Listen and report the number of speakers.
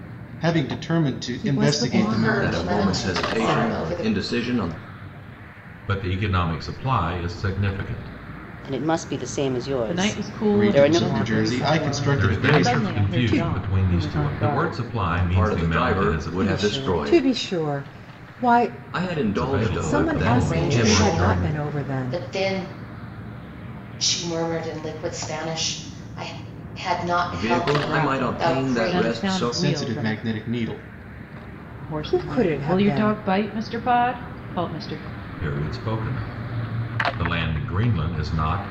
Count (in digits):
7